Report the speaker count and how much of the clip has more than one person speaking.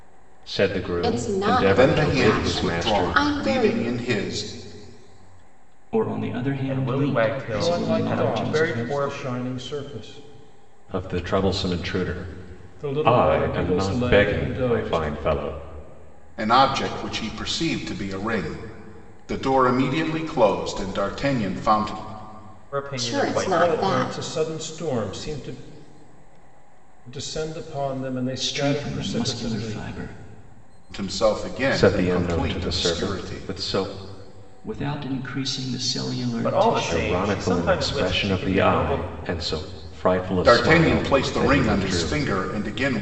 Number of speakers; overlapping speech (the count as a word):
six, about 39%